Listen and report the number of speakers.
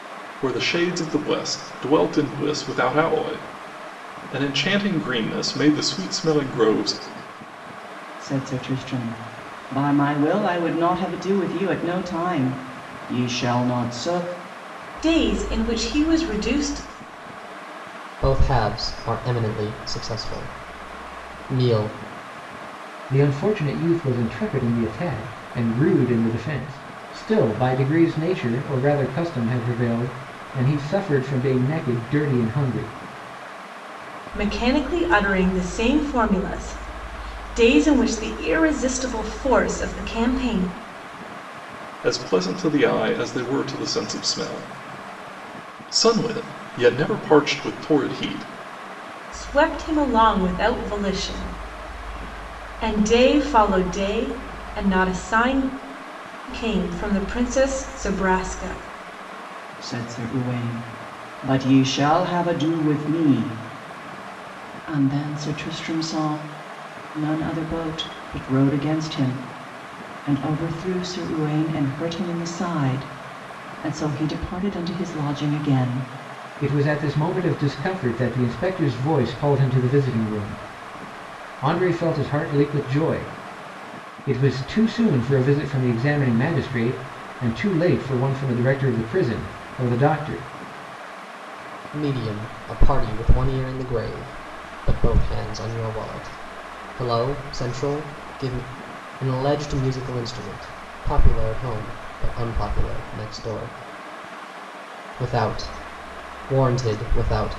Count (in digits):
5